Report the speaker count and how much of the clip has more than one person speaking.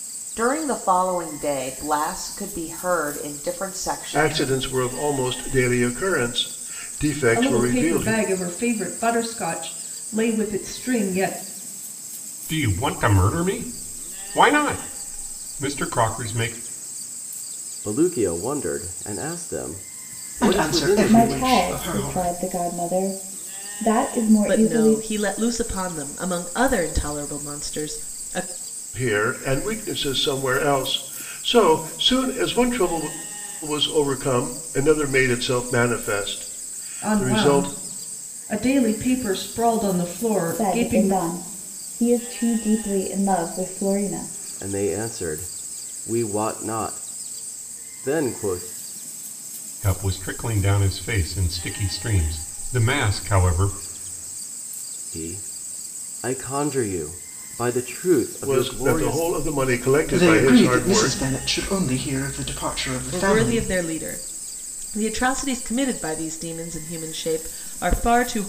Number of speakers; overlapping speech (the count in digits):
8, about 12%